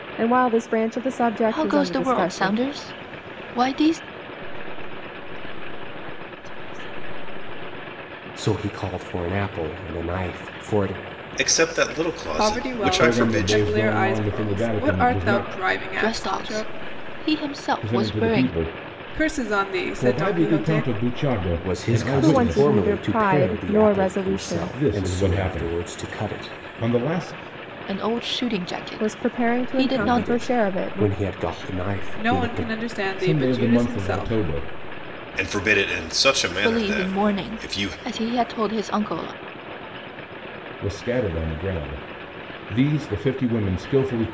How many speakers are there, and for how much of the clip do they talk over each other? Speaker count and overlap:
seven, about 43%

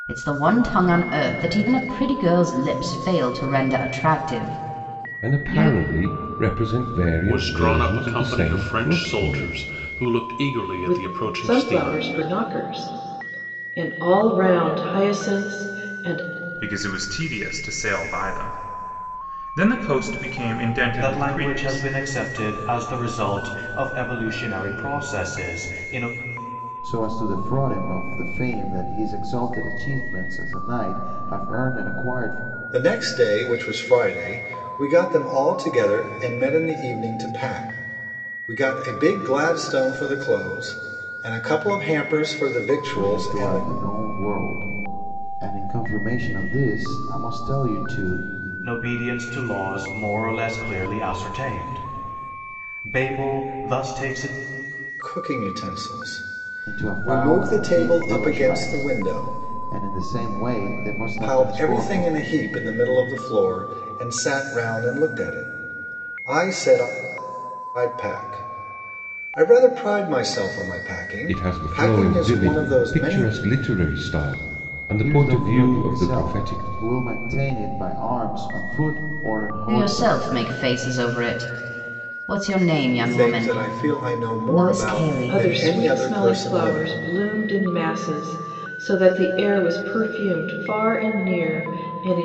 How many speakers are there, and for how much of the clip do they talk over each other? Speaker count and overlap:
eight, about 20%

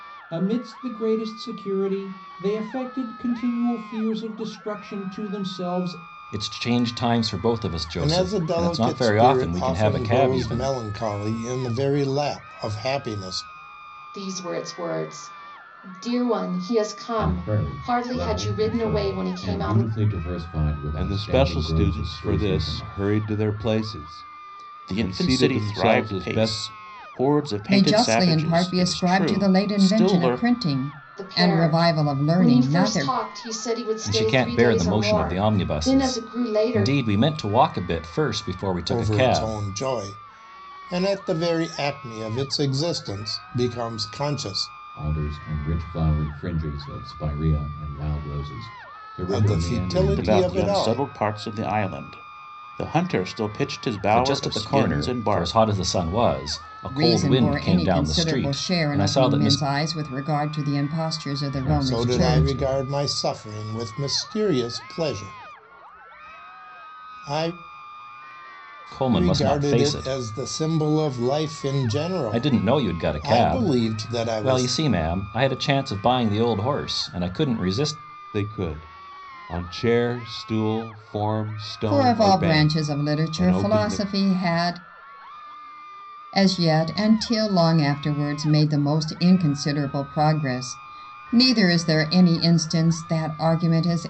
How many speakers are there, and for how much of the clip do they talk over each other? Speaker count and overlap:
eight, about 33%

